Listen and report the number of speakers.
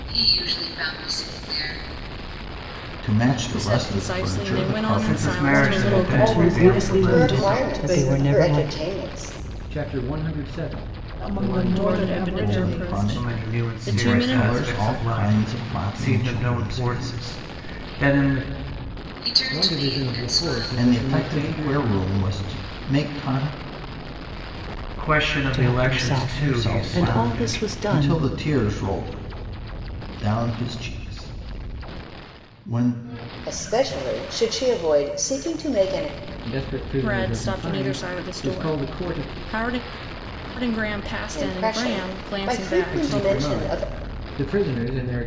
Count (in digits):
8